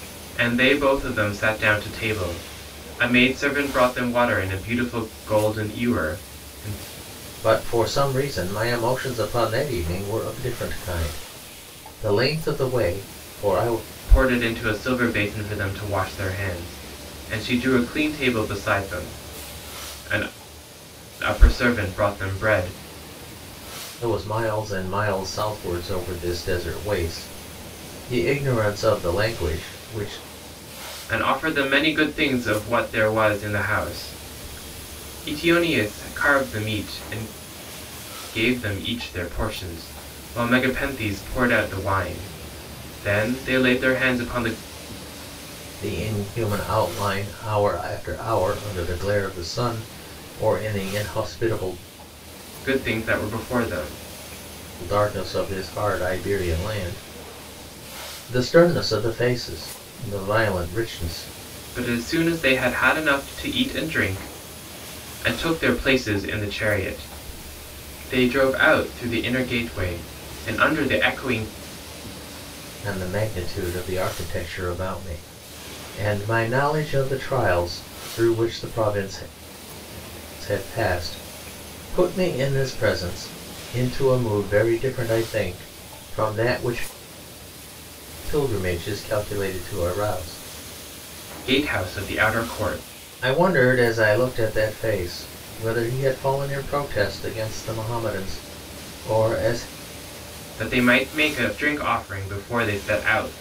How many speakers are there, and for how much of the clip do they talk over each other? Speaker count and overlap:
two, no overlap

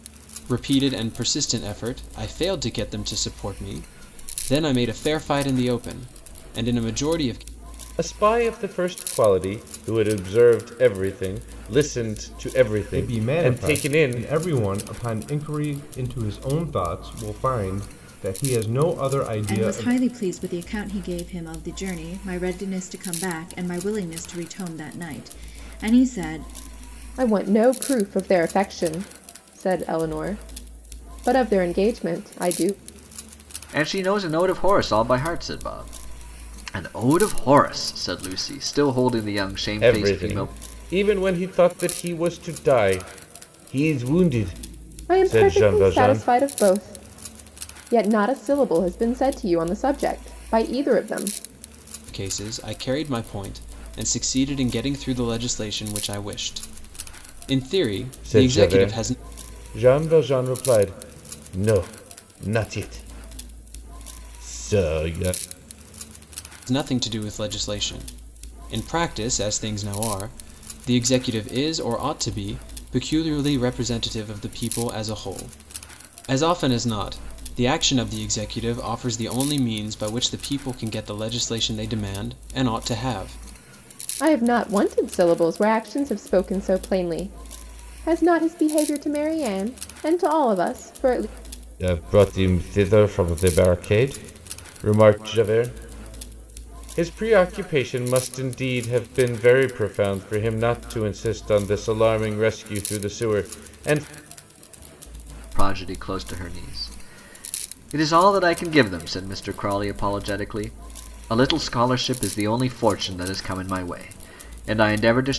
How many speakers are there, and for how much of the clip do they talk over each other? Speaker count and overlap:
six, about 4%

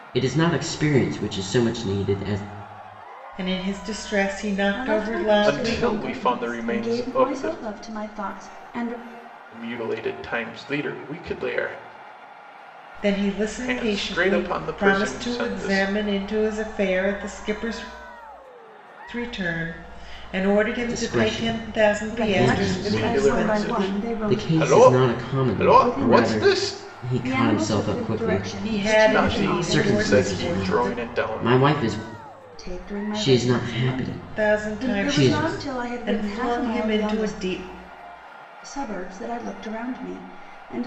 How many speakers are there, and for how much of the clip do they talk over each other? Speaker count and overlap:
four, about 46%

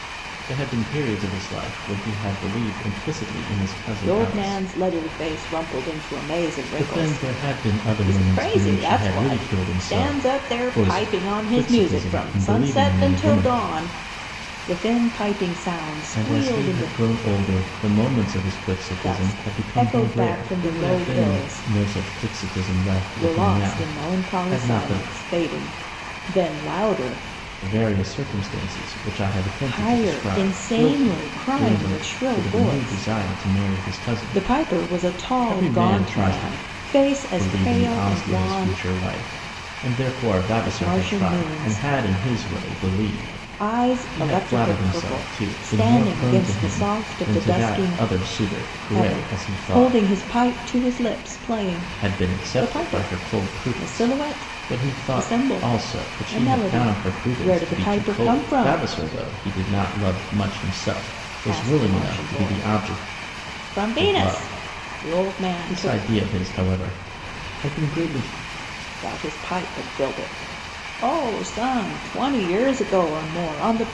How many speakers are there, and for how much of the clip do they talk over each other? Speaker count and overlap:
two, about 49%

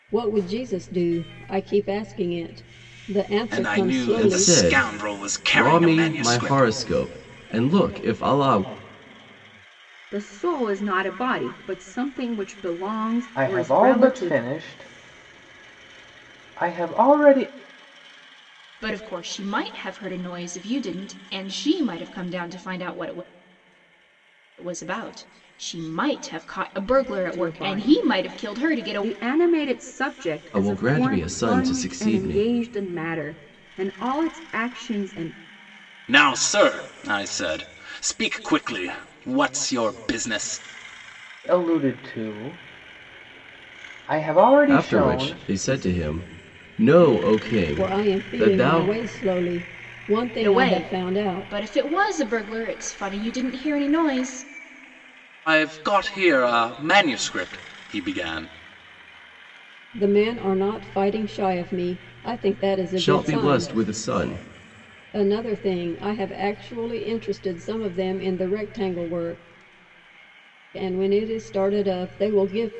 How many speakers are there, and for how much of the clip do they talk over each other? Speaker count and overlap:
six, about 17%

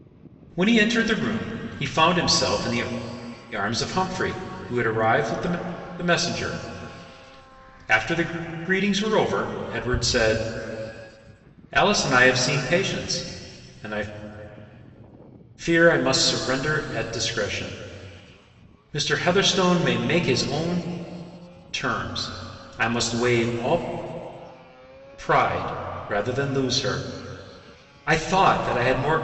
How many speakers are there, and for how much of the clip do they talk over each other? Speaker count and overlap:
one, no overlap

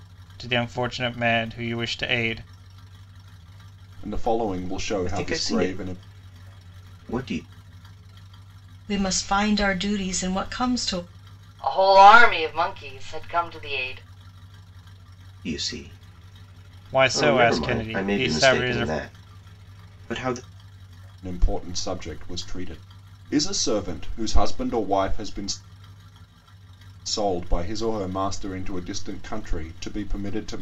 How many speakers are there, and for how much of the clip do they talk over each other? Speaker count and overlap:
five, about 10%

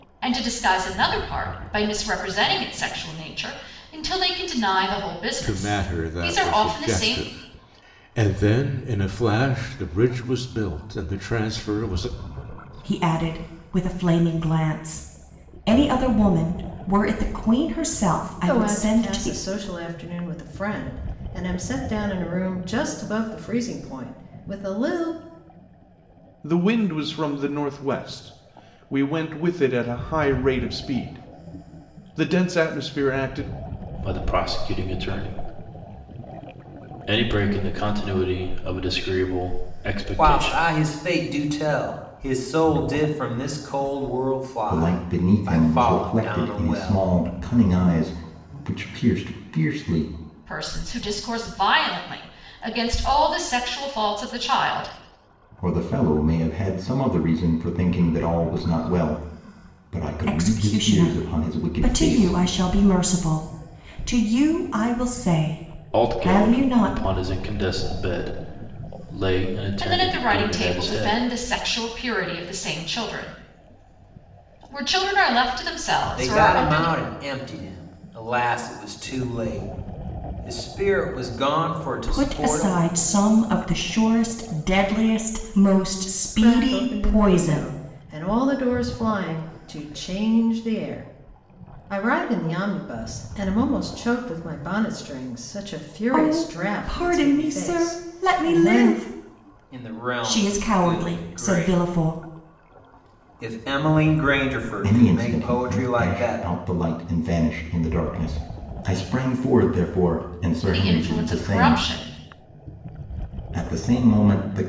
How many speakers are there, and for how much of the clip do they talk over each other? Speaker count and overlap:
eight, about 19%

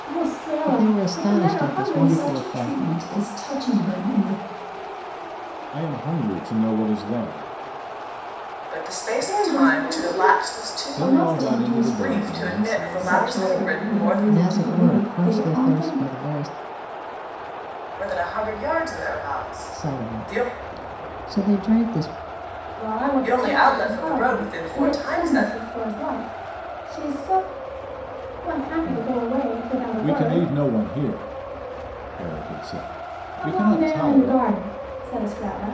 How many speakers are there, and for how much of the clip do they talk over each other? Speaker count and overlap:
five, about 42%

